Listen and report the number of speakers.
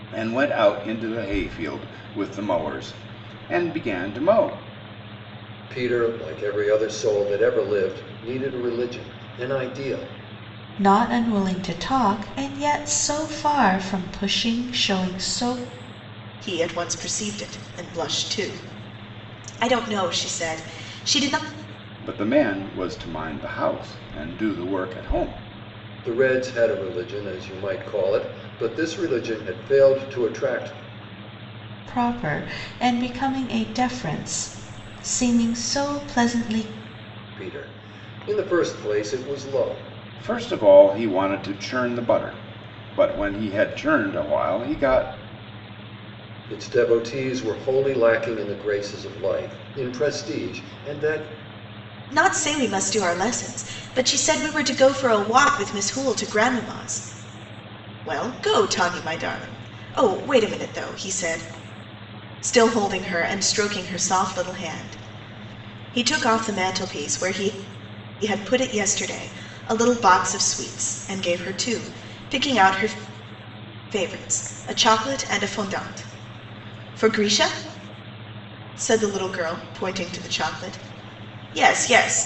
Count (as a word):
four